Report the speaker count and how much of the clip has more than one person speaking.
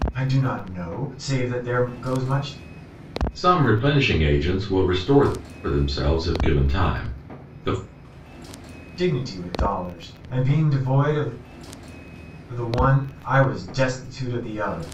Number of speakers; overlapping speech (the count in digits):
2, no overlap